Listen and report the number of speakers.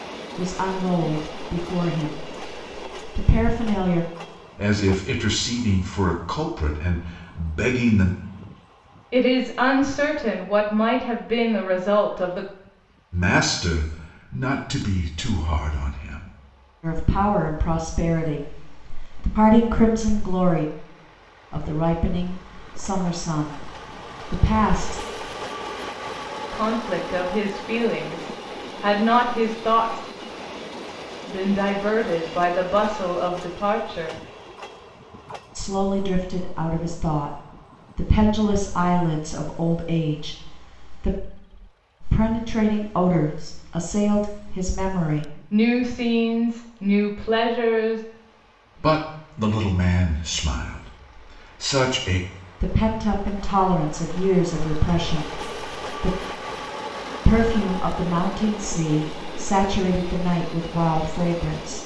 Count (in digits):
3